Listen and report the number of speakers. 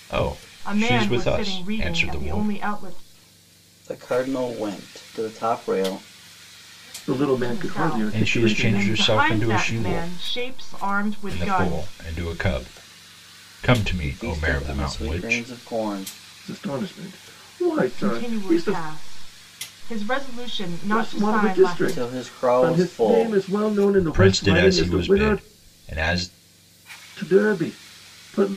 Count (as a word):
four